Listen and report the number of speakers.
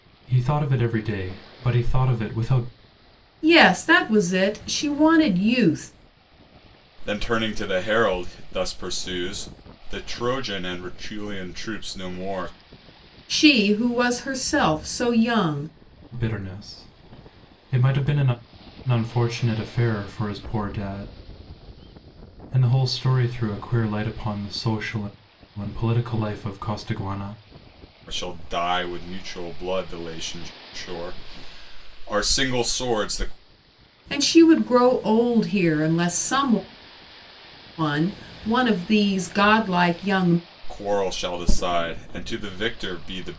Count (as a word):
three